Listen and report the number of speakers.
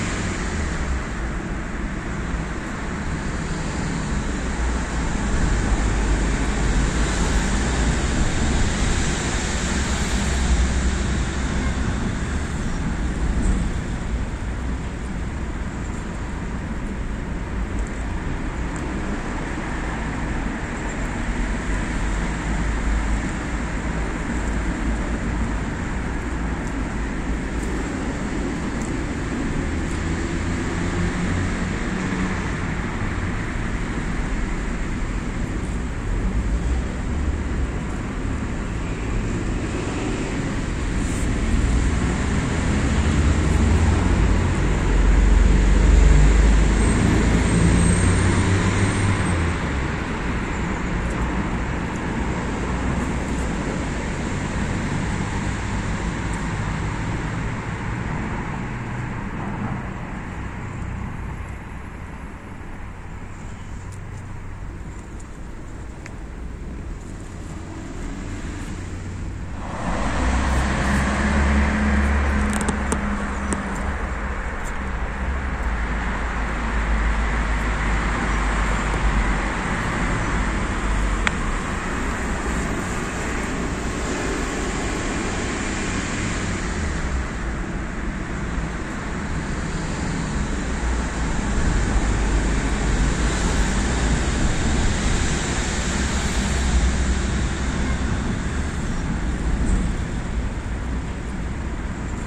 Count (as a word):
zero